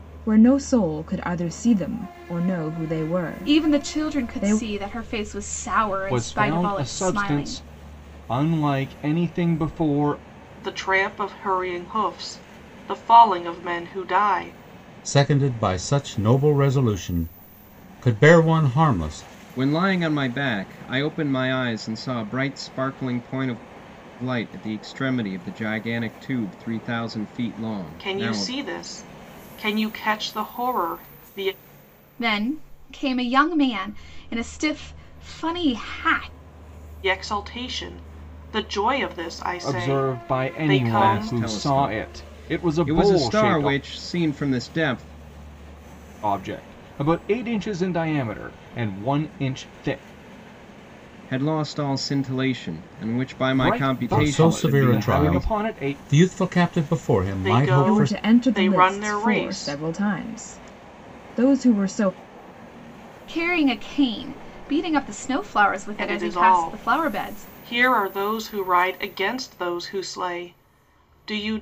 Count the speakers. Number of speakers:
six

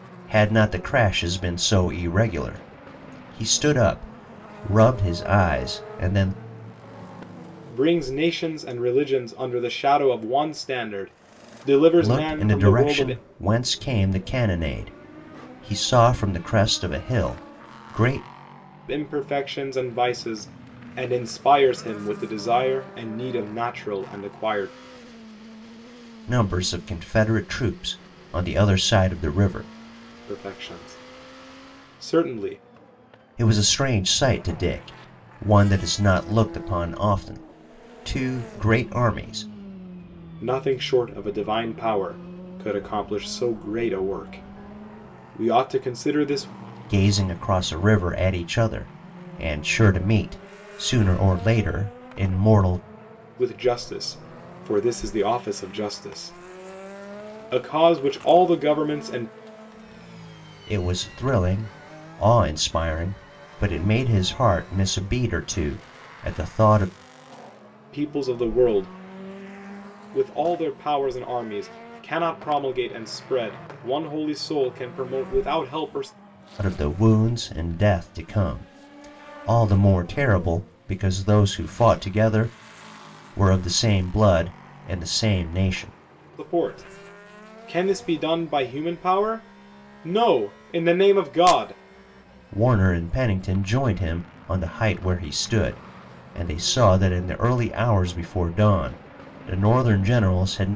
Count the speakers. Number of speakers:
two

